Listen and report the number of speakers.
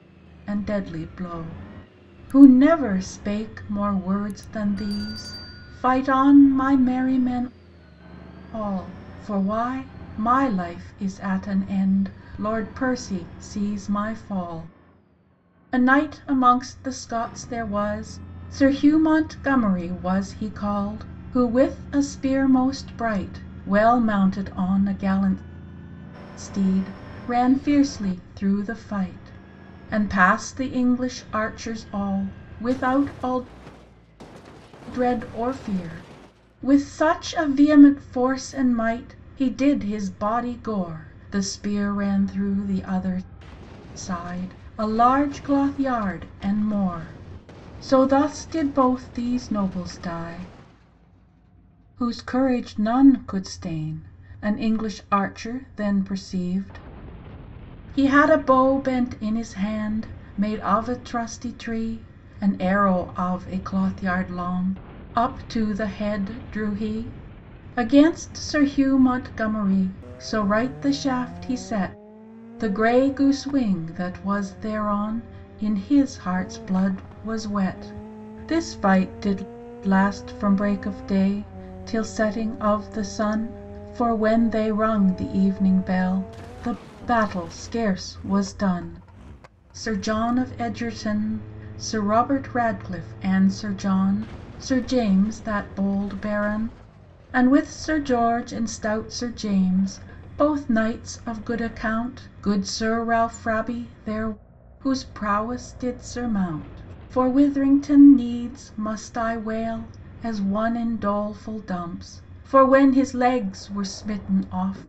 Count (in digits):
1